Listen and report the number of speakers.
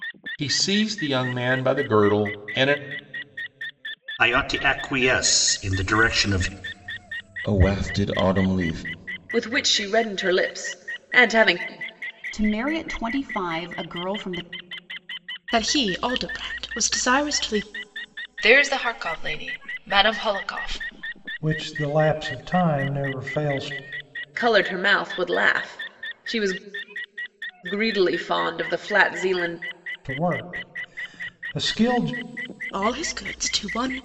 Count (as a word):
eight